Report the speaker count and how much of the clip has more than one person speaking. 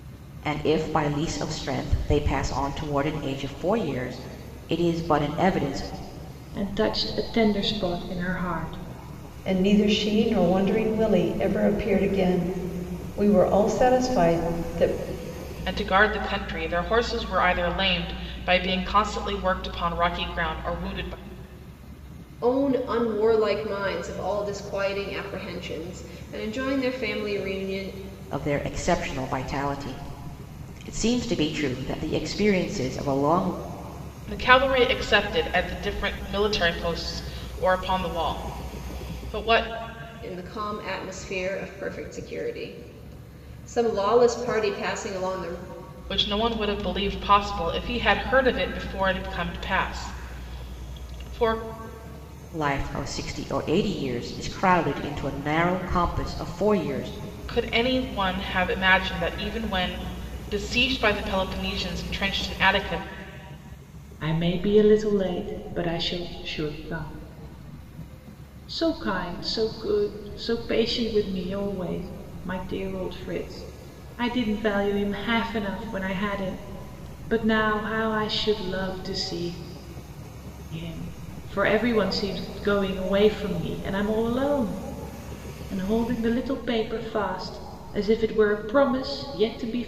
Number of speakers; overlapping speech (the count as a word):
five, no overlap